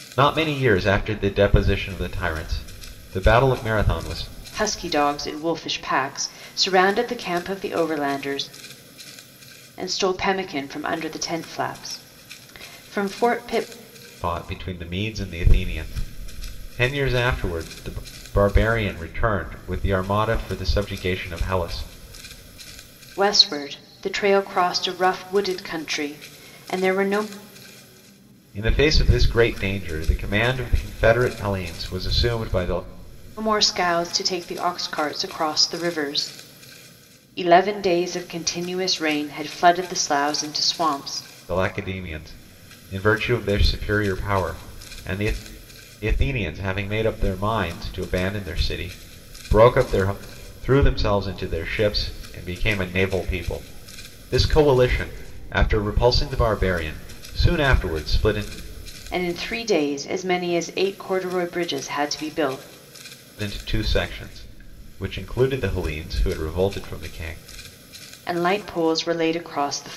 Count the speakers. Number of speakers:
2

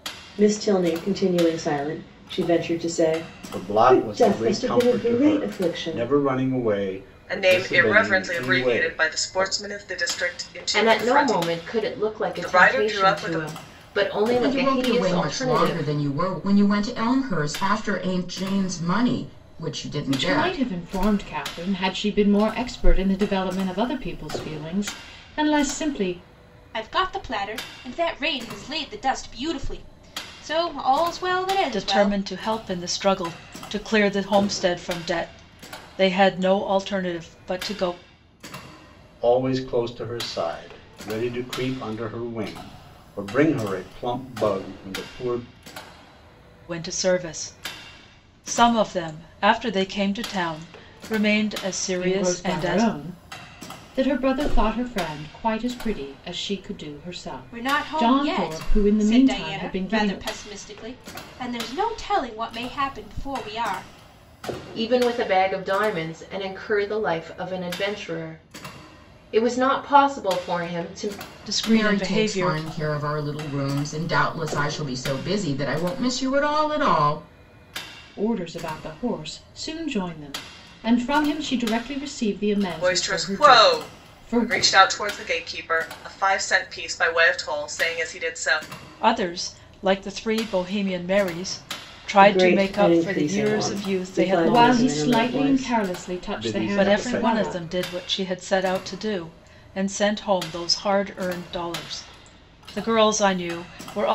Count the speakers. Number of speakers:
8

